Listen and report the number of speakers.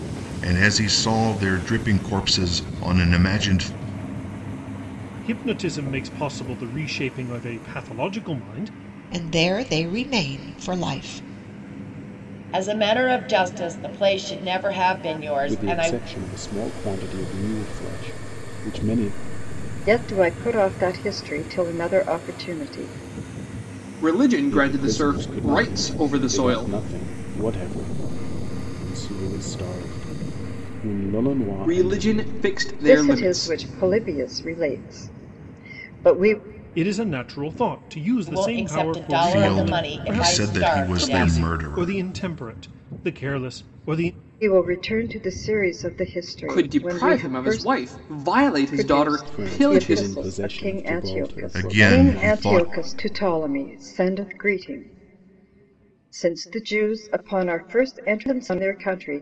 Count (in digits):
7